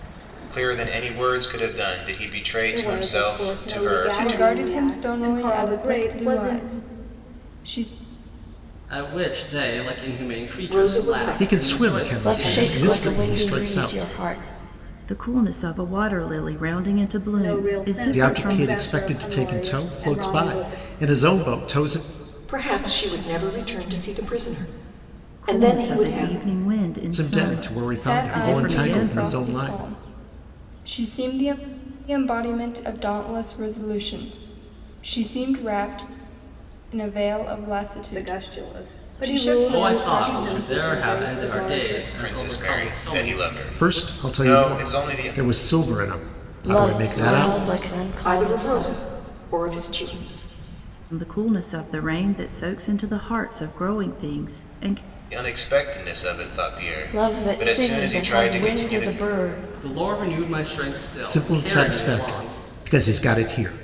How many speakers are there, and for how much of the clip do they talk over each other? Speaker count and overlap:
eight, about 44%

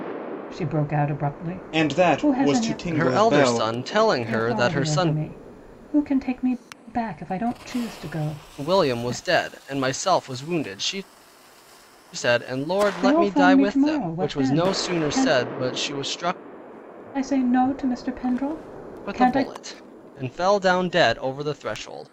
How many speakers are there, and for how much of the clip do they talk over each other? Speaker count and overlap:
three, about 29%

